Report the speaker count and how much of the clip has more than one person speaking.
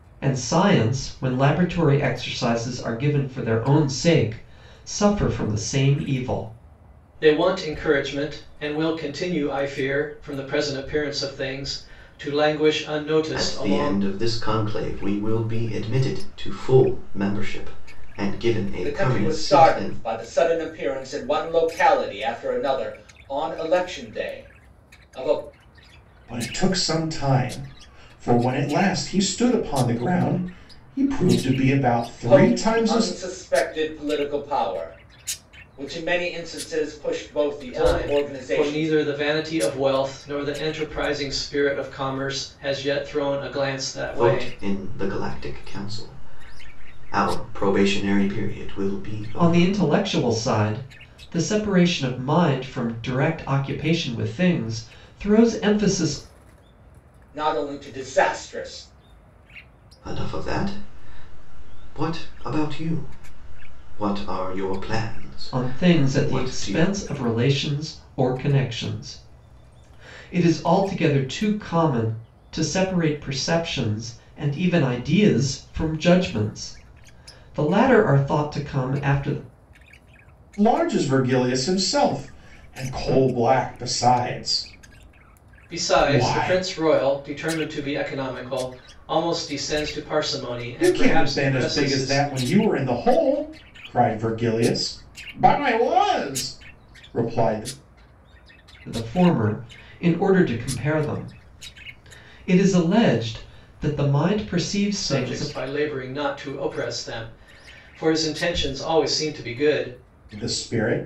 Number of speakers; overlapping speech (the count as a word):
five, about 8%